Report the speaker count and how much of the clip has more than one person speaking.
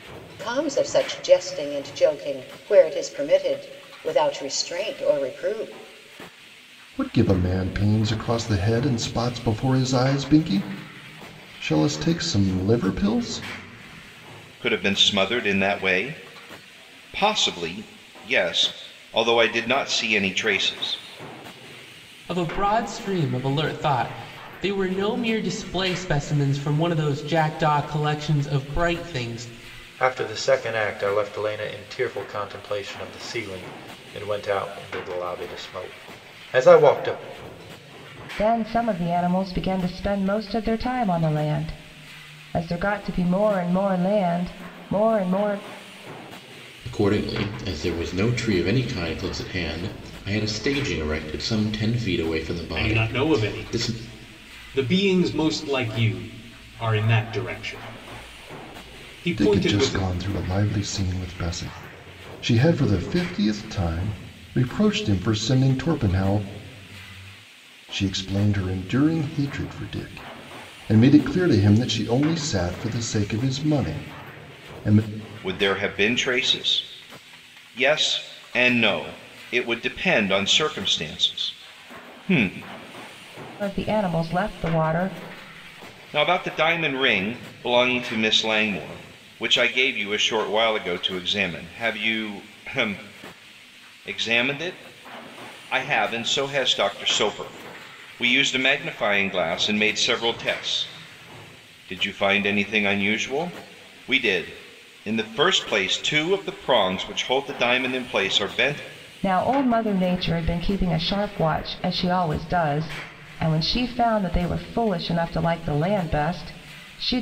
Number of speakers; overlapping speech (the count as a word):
eight, about 2%